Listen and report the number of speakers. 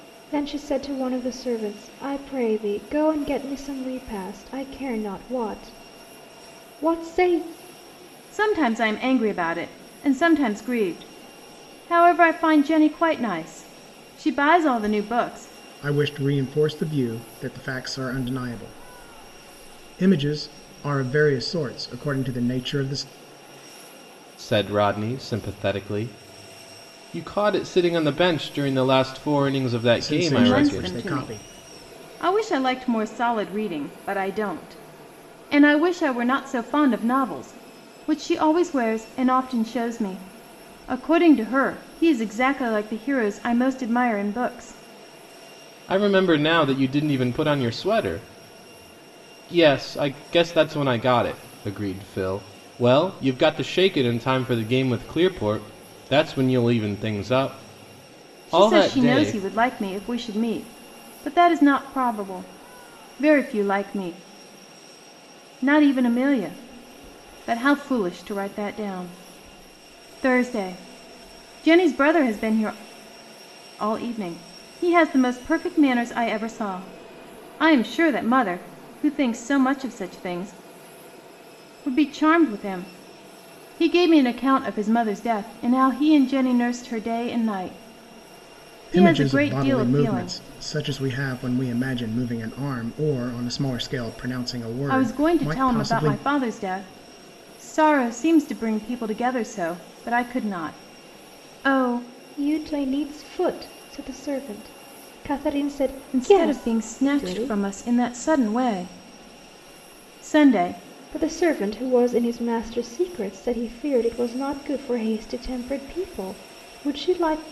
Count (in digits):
4